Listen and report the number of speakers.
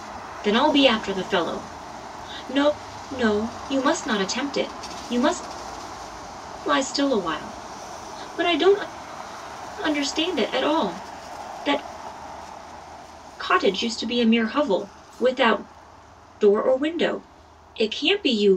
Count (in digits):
1